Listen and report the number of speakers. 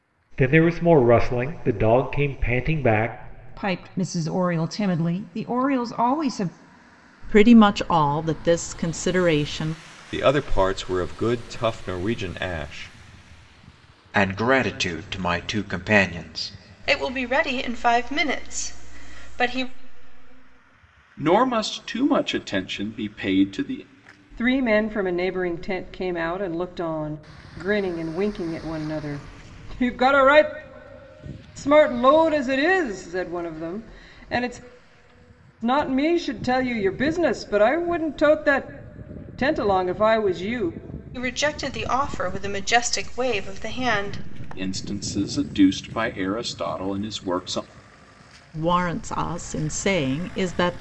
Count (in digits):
8